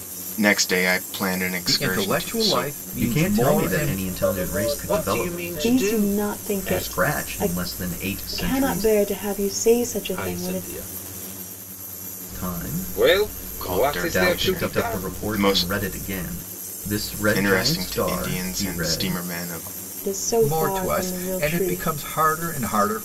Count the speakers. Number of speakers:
6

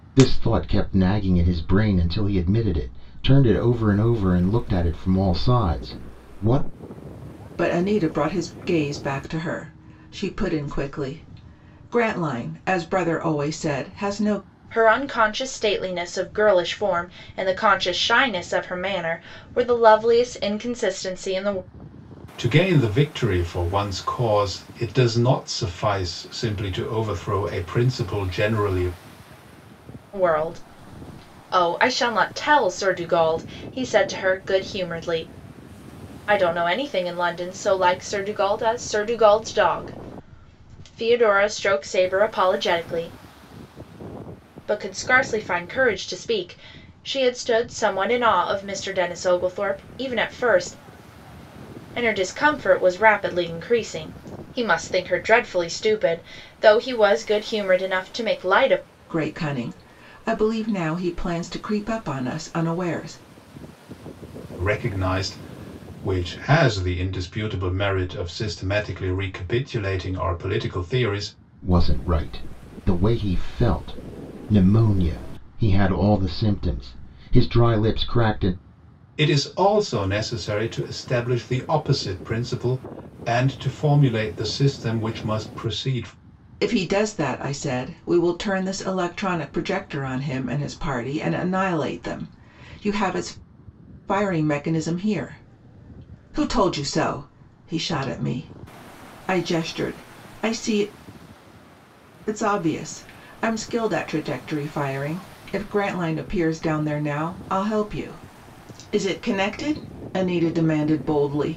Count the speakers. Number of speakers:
4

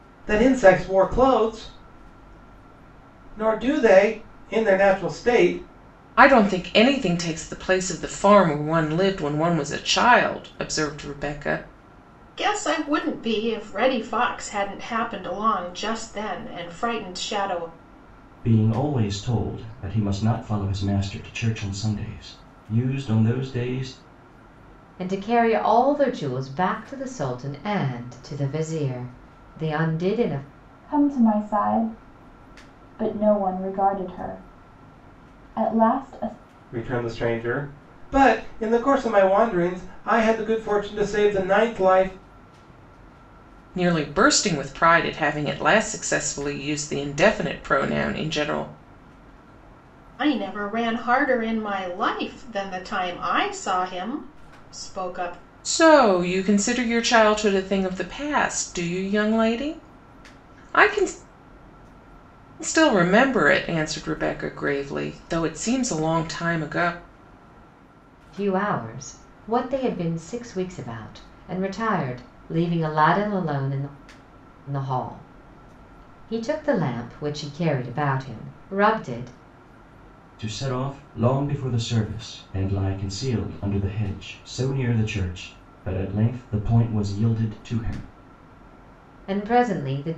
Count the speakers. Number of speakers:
6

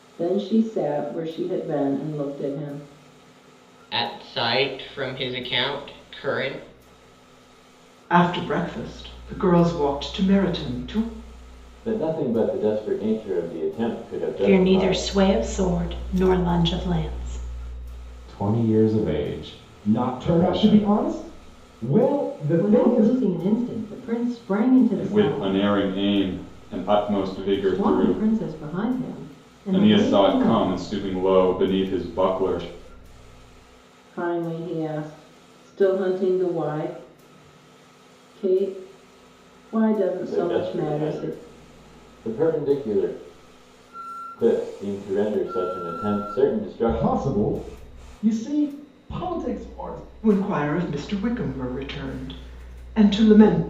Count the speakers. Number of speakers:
9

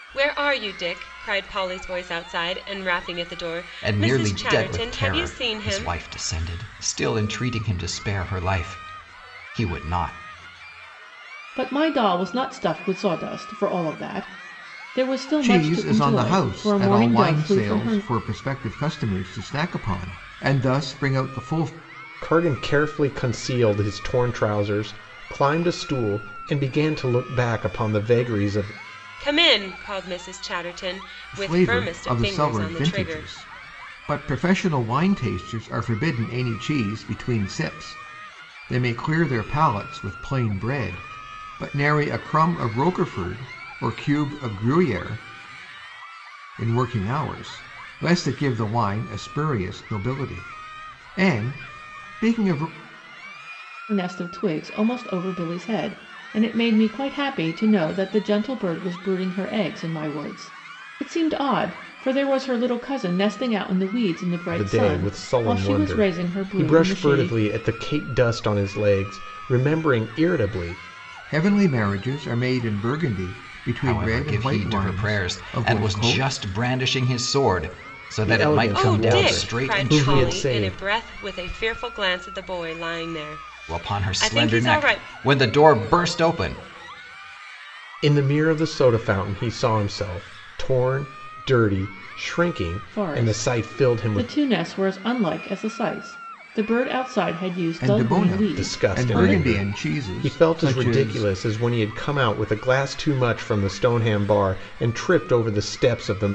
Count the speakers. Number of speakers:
5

